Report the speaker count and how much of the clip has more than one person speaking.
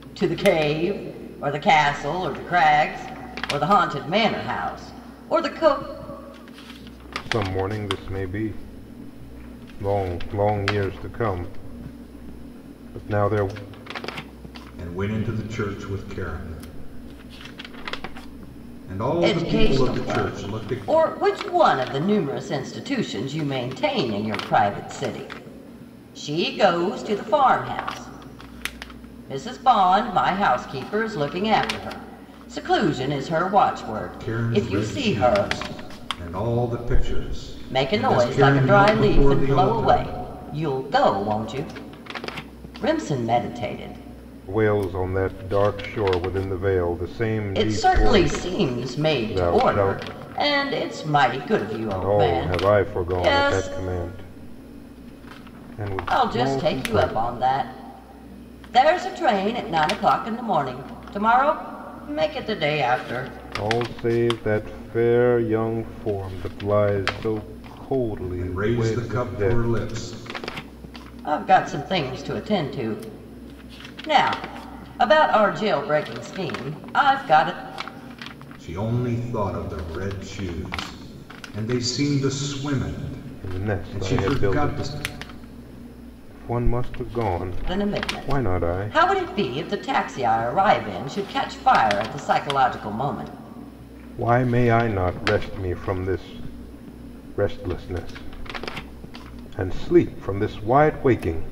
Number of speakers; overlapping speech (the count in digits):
3, about 15%